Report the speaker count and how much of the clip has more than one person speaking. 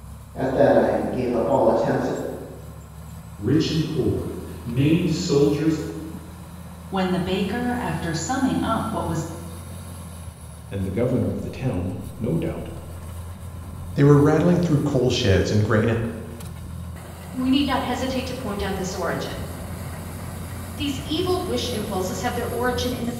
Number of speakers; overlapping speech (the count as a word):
six, no overlap